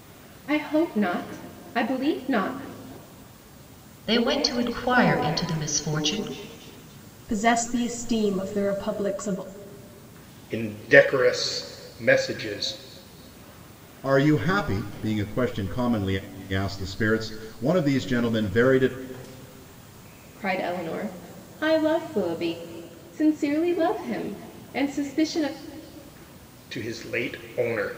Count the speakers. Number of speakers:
5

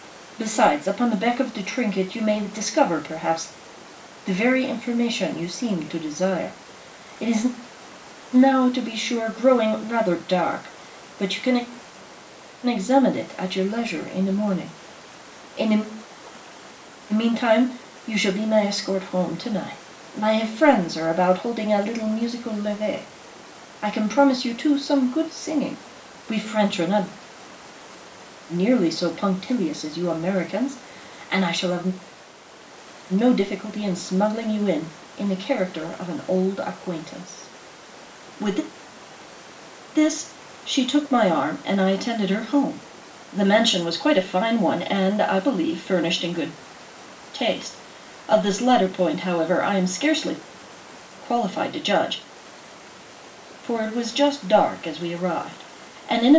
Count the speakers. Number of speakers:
1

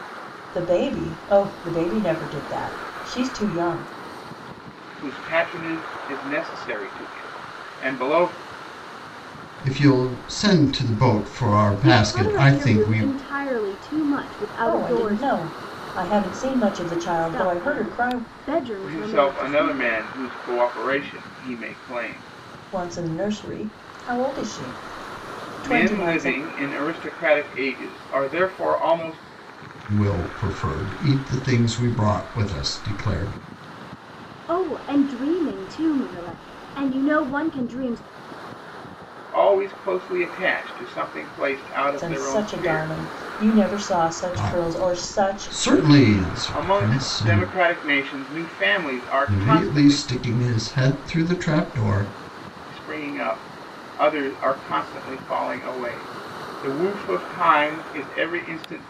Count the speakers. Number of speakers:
4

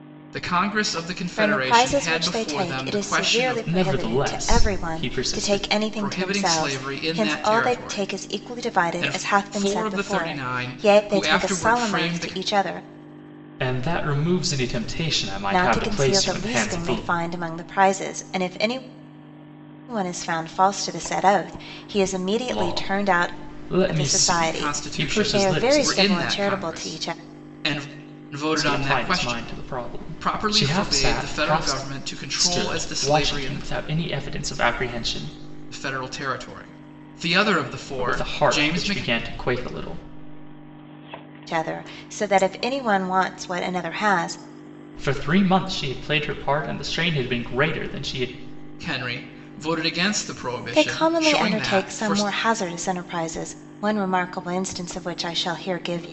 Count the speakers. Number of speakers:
3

